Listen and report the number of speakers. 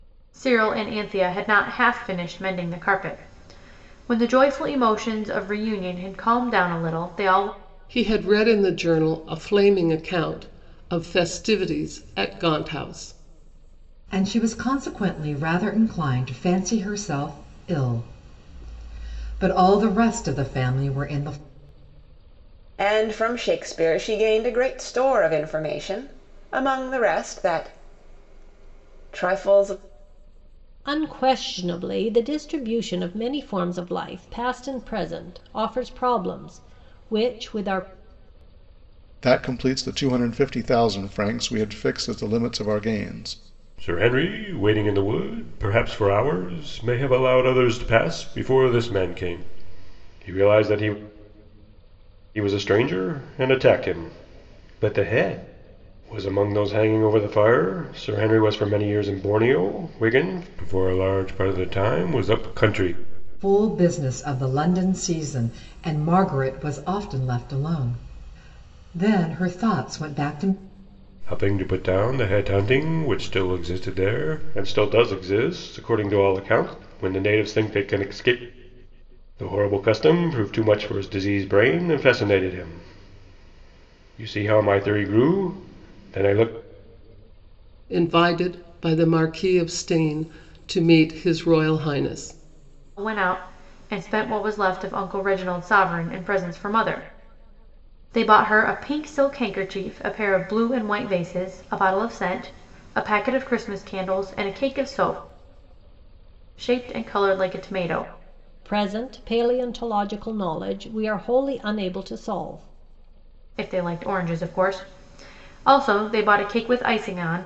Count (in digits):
7